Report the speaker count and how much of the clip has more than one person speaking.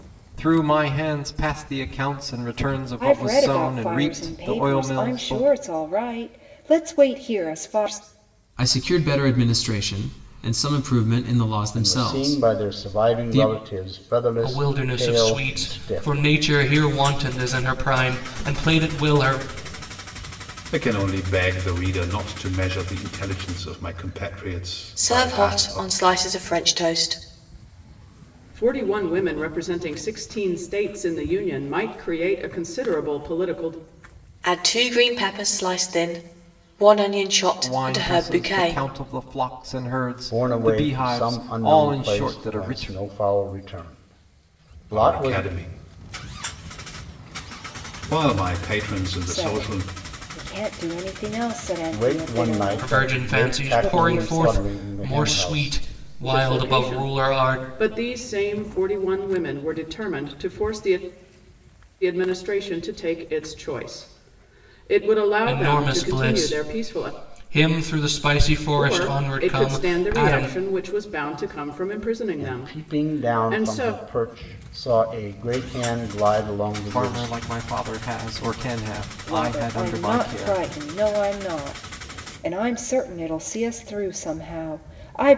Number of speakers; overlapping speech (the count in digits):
8, about 29%